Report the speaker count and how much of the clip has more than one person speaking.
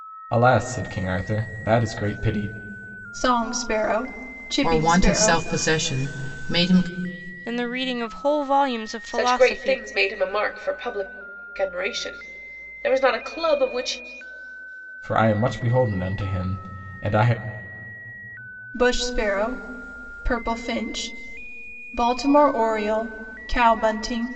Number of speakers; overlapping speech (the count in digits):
5, about 6%